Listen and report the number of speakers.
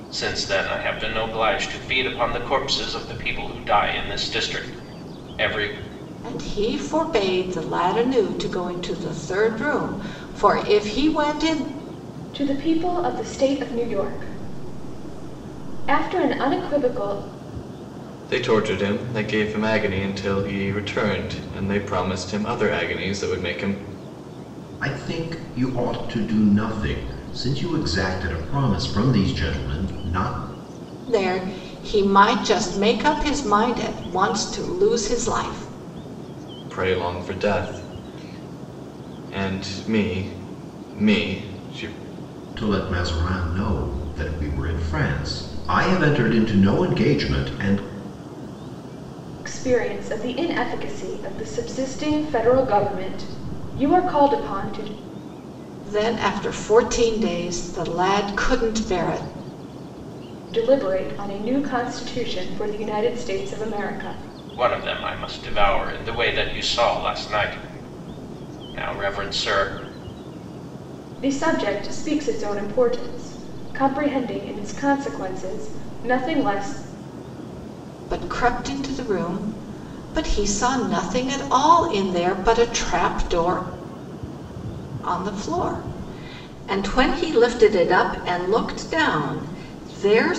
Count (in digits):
5